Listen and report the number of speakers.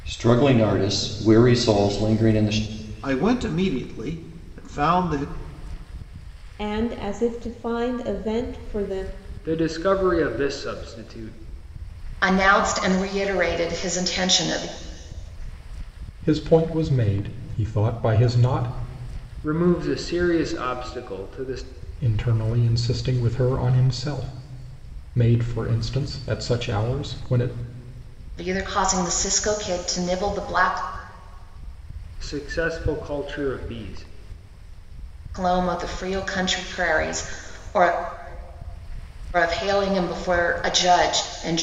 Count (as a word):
six